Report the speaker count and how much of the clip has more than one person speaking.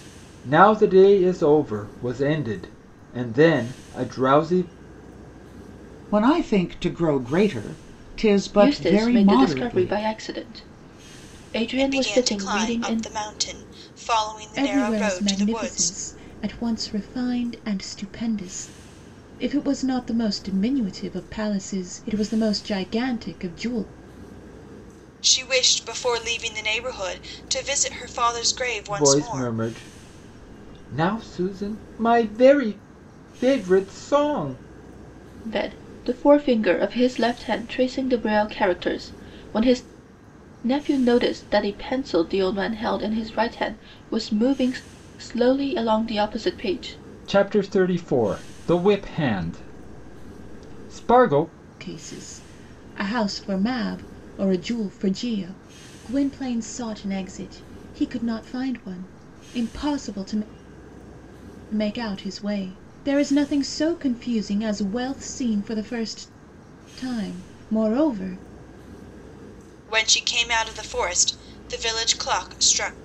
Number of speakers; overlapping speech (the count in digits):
5, about 7%